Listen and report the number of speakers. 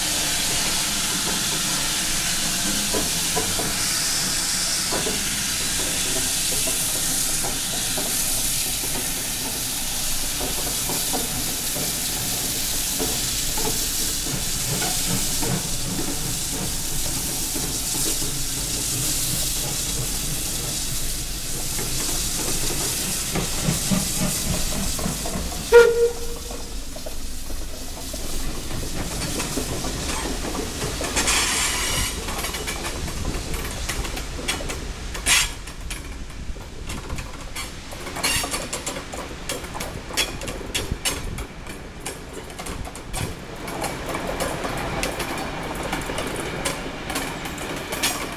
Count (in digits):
0